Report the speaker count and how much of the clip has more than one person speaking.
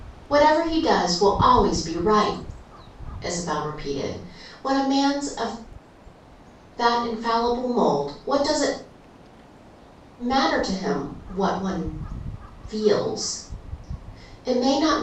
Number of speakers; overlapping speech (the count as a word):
one, no overlap